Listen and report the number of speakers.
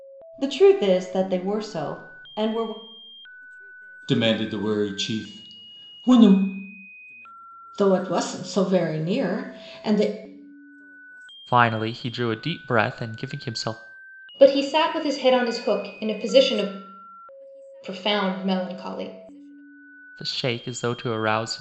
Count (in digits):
5